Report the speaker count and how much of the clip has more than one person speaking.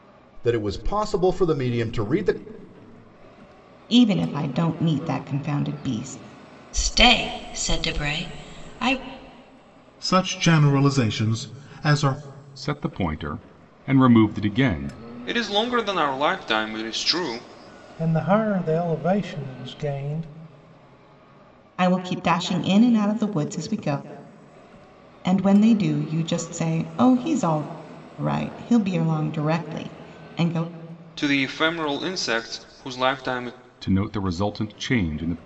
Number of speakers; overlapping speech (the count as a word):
seven, no overlap